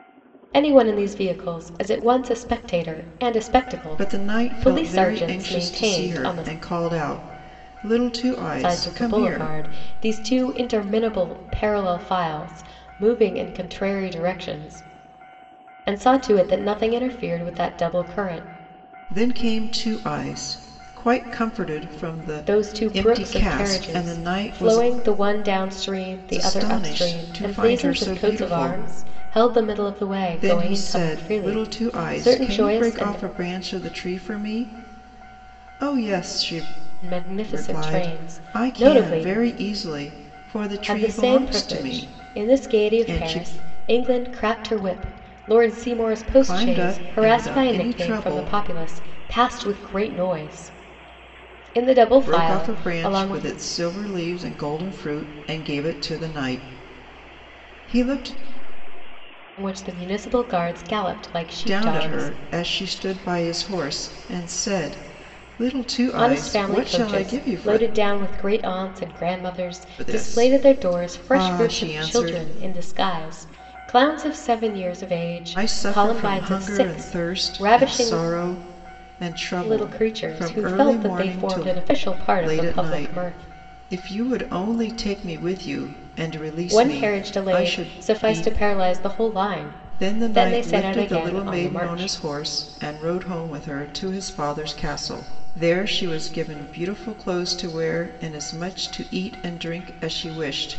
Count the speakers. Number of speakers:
two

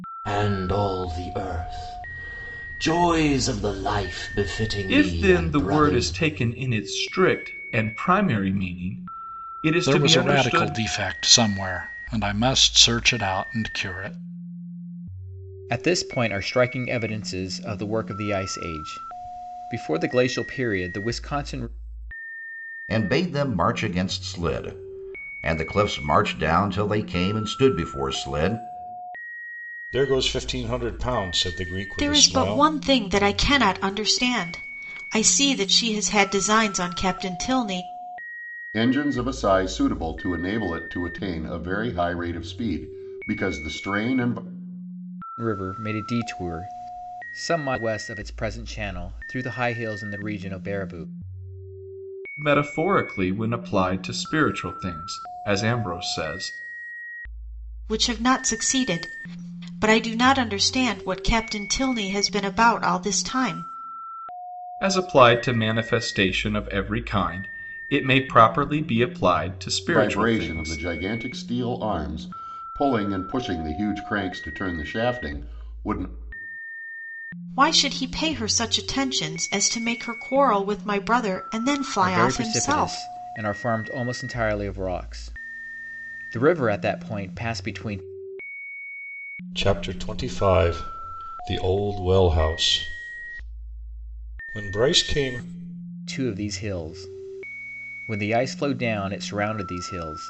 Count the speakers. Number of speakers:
eight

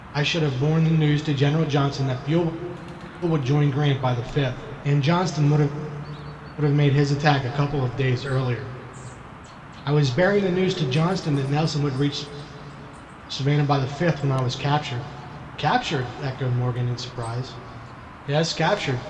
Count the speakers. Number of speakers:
one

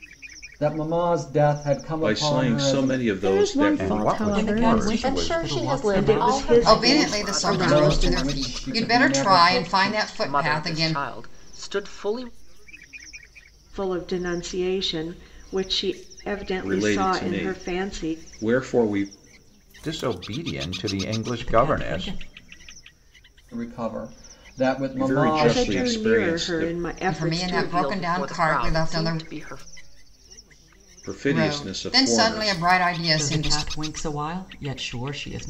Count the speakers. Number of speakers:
nine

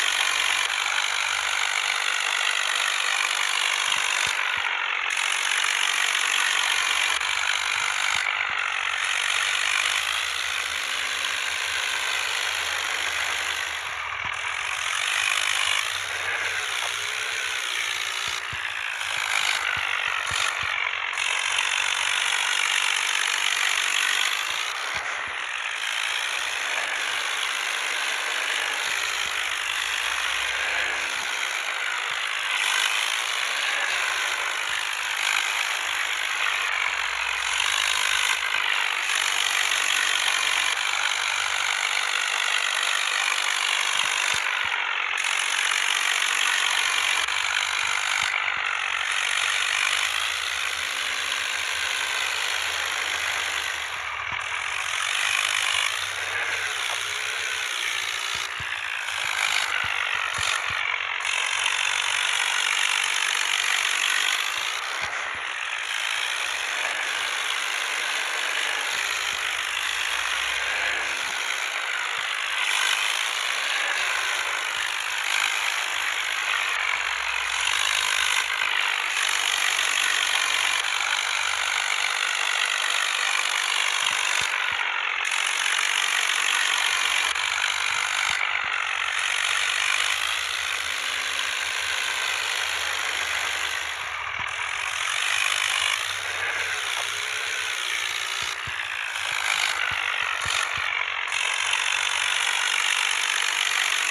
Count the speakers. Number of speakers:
zero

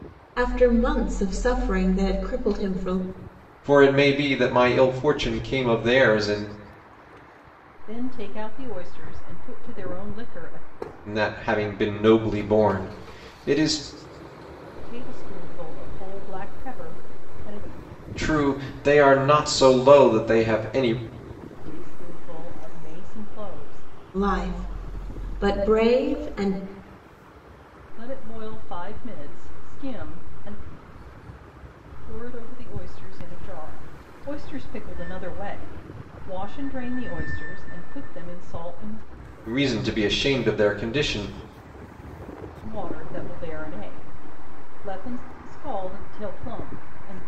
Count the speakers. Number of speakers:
three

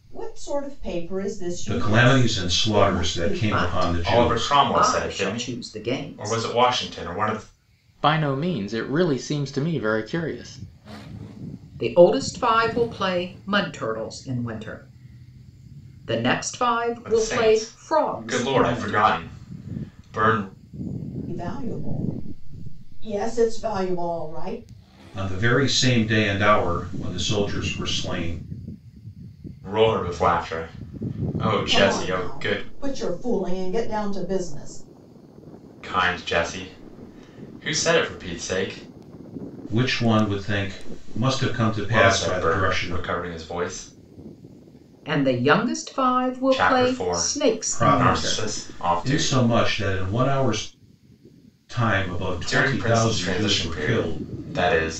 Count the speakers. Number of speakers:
five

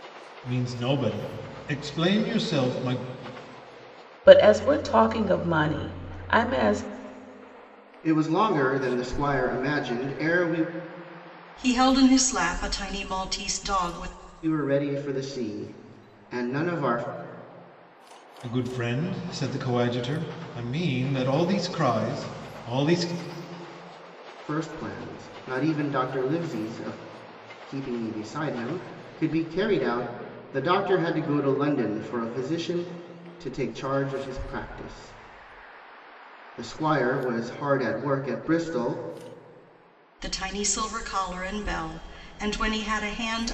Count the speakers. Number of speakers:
four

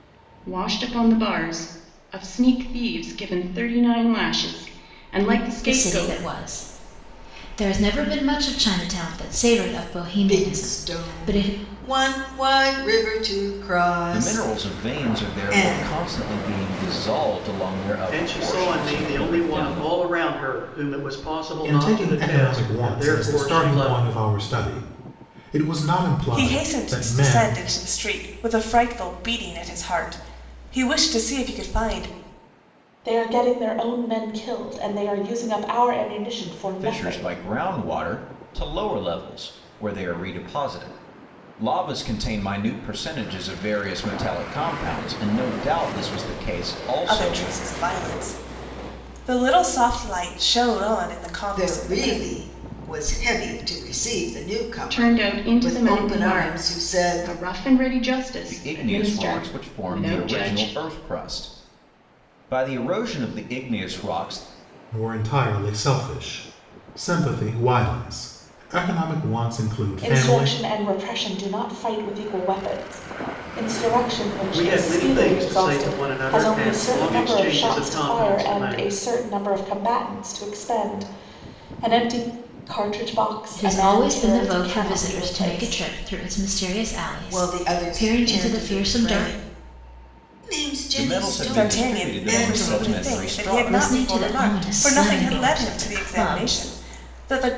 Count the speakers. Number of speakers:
eight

